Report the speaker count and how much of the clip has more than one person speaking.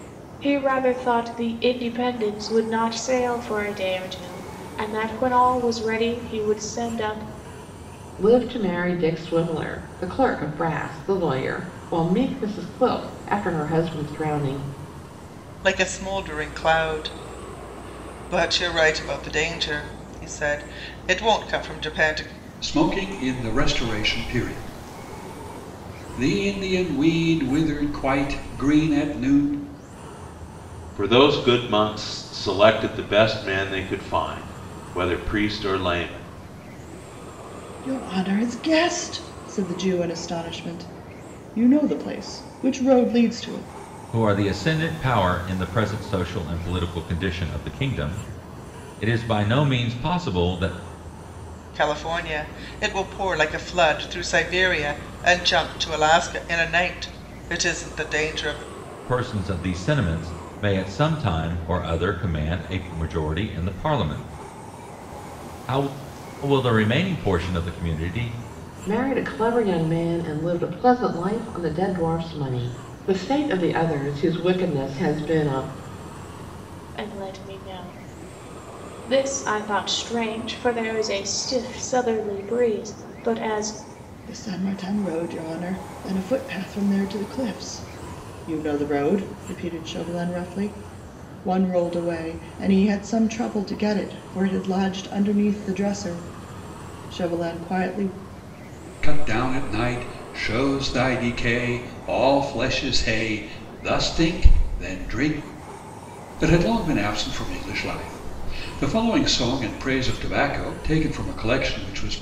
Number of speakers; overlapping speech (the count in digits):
7, no overlap